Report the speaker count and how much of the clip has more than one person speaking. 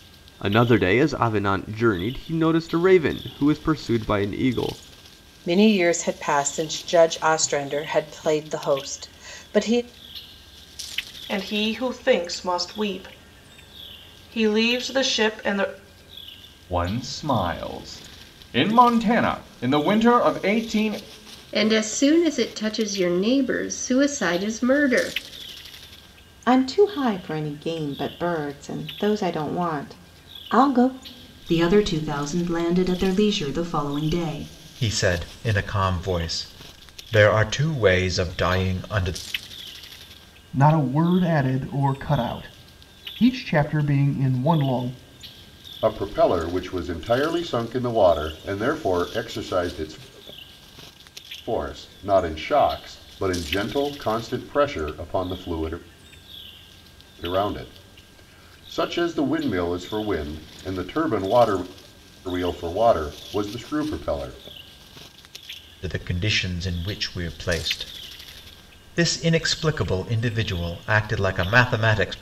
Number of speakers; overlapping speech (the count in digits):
10, no overlap